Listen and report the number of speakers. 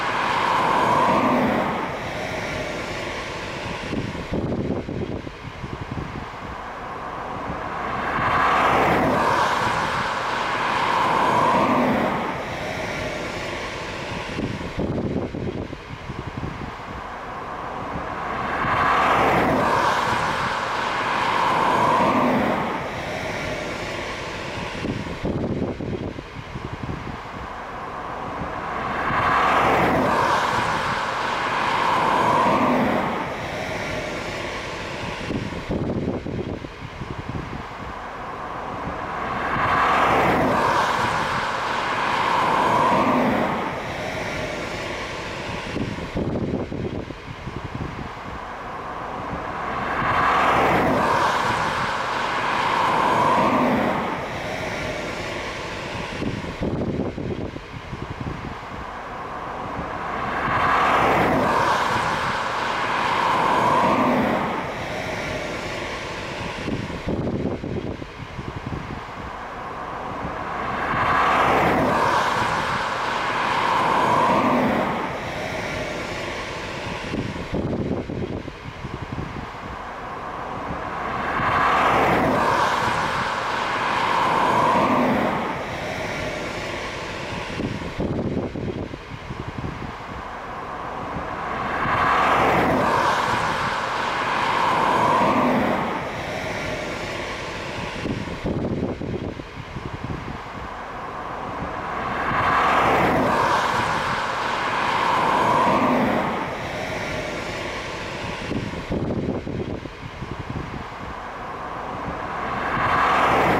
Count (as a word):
zero